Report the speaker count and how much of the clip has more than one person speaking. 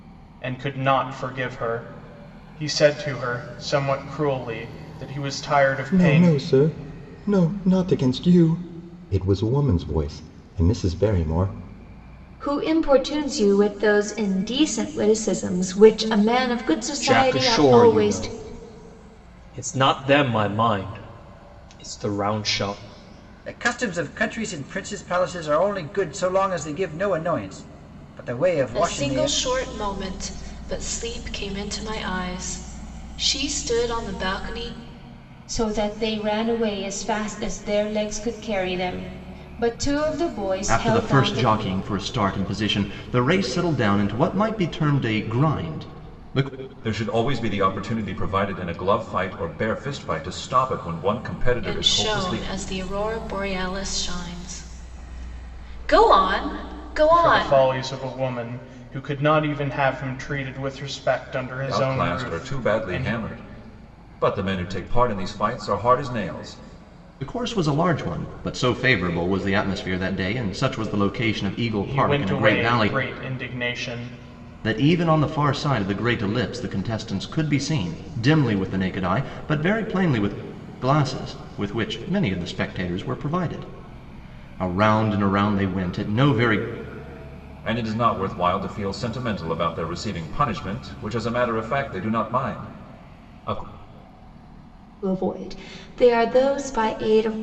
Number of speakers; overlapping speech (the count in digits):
9, about 7%